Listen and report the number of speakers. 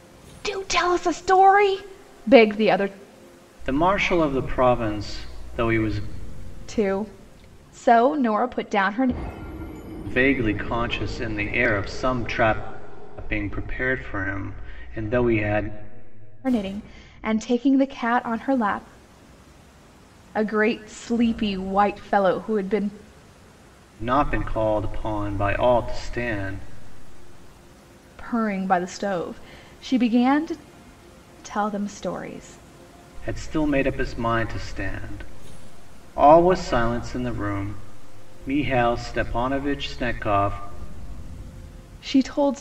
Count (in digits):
2